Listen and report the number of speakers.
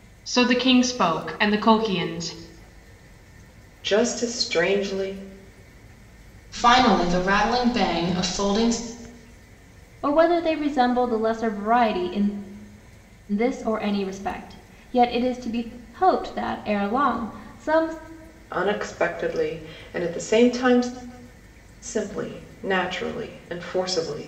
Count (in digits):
4